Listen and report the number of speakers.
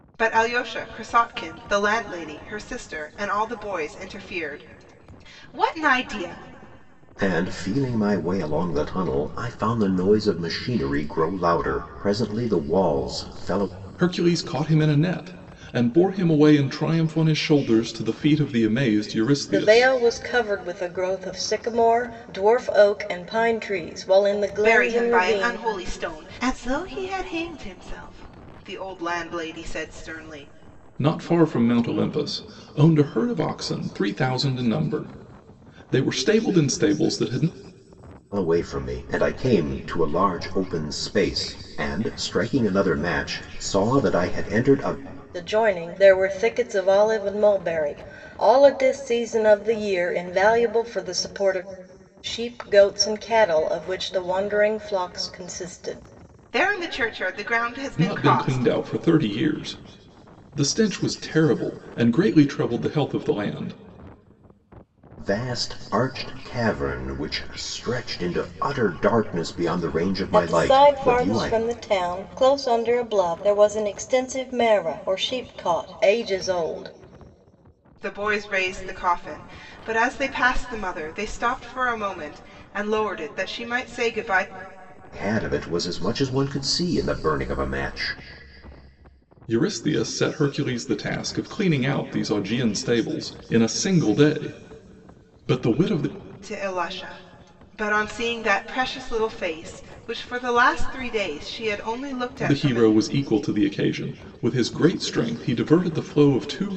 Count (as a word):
four